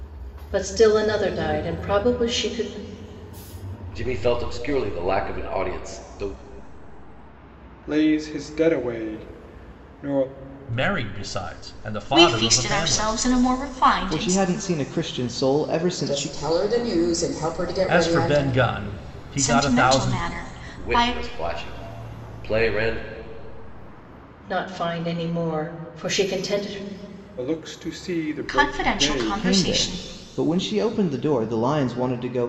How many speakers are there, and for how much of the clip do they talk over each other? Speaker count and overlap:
7, about 16%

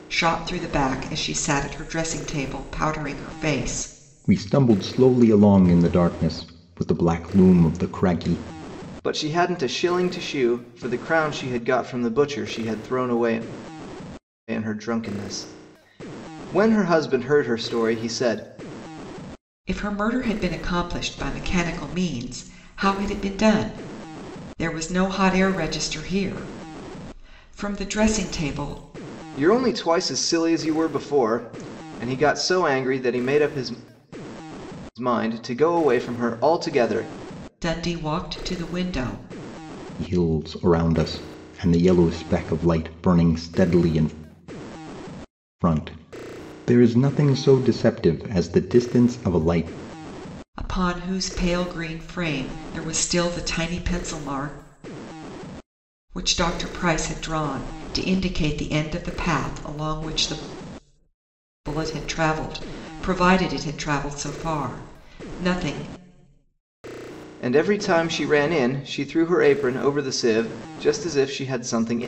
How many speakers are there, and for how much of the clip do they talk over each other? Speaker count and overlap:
3, no overlap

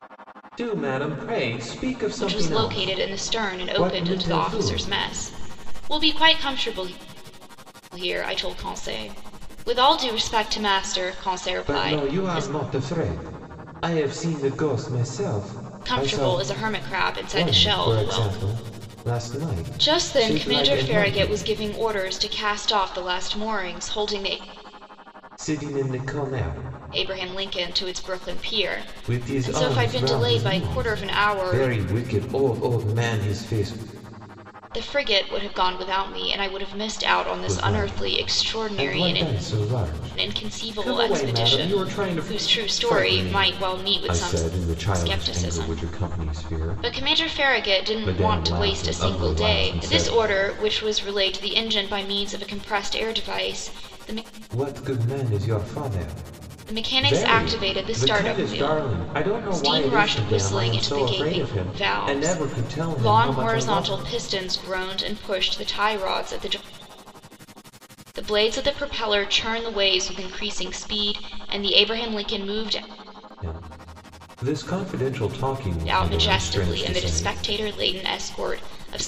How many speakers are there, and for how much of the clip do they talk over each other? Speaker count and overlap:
2, about 35%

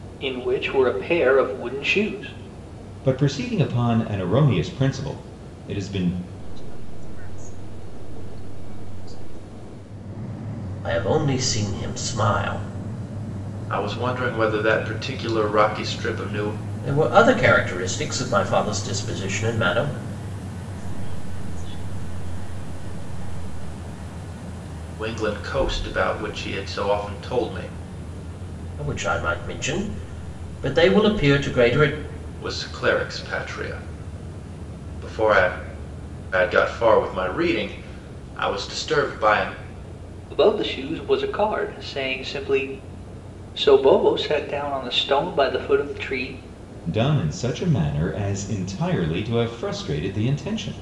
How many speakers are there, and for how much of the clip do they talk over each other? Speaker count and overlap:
5, no overlap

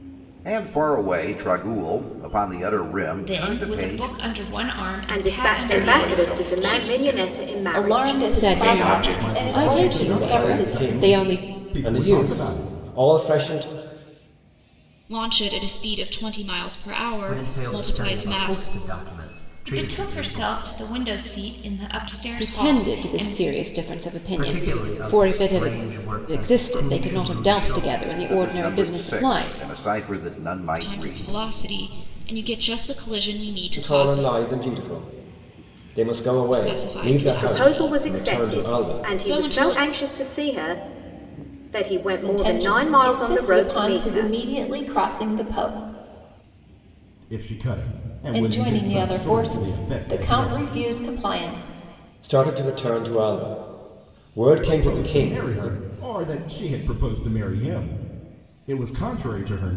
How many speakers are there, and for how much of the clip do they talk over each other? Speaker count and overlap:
10, about 45%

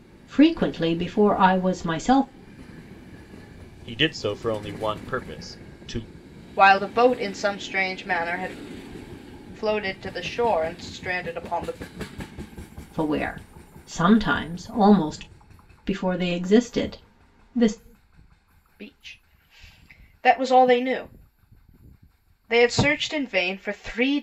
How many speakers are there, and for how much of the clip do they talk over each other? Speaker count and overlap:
3, no overlap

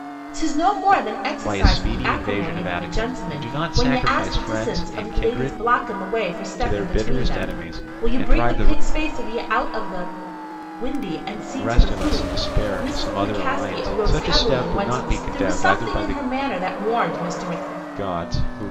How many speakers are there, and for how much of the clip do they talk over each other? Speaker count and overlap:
2, about 57%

